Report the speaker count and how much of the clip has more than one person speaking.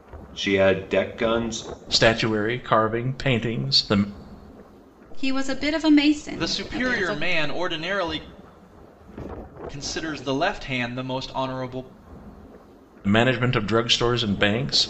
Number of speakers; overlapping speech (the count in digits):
4, about 6%